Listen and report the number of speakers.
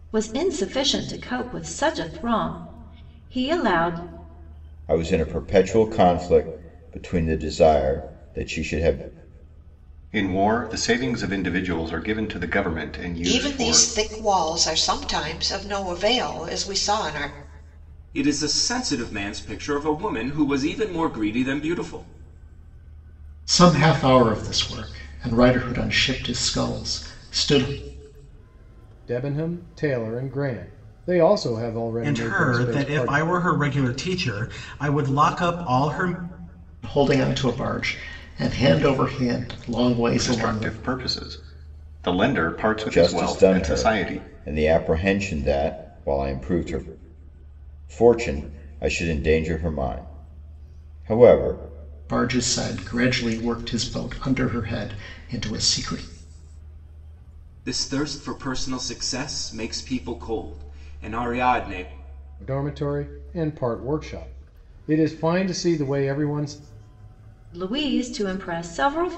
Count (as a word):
eight